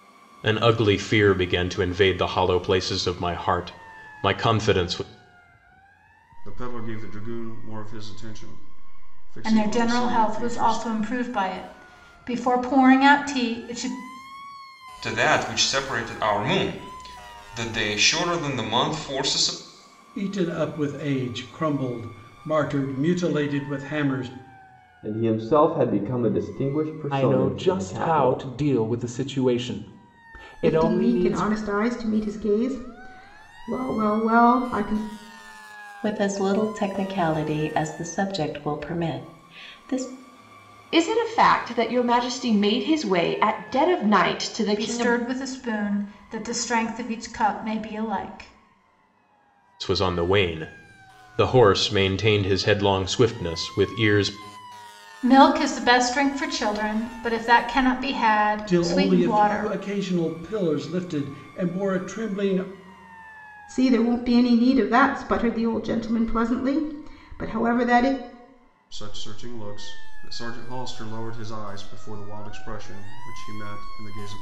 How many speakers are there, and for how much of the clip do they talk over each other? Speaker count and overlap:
10, about 7%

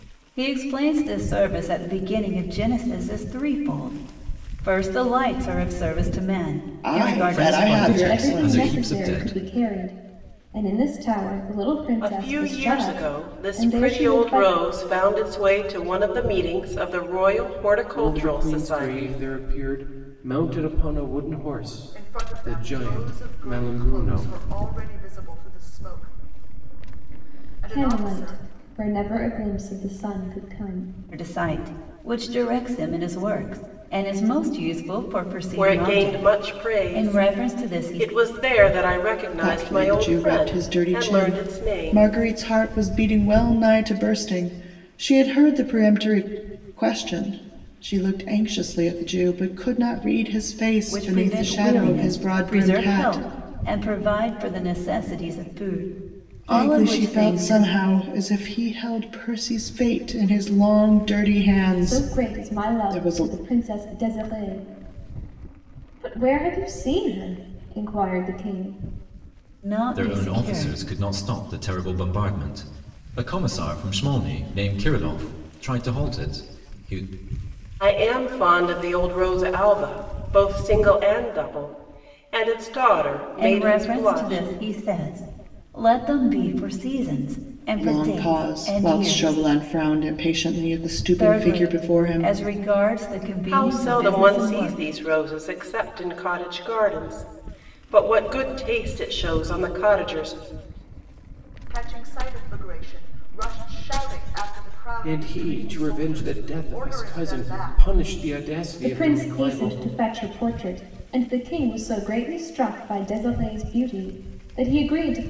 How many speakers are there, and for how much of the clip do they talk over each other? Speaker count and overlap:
7, about 26%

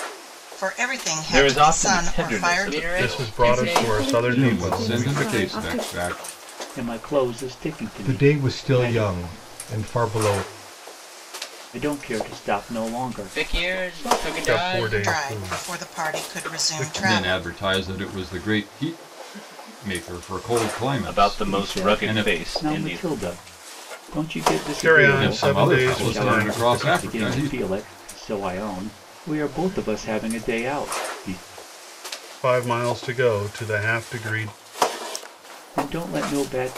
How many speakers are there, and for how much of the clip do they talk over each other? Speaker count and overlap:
8, about 39%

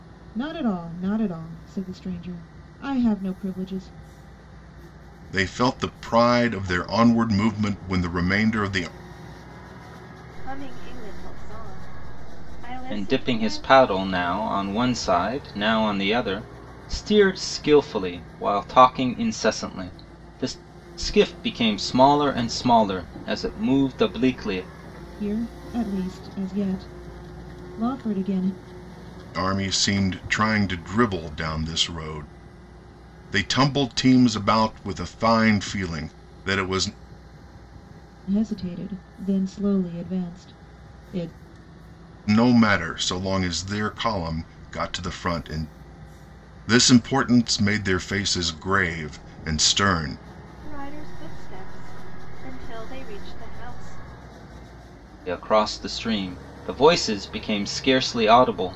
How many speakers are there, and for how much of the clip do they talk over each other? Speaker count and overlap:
4, about 1%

